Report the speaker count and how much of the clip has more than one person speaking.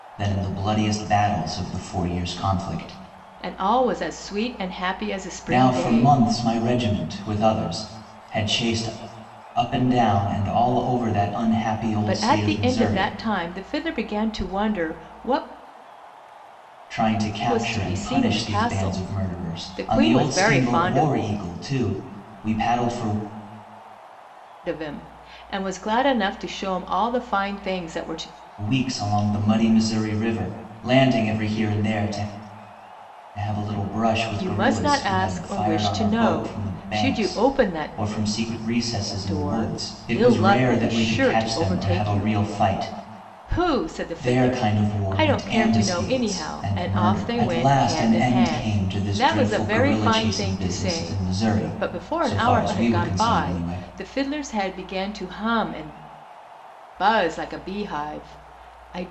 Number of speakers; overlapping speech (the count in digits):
2, about 36%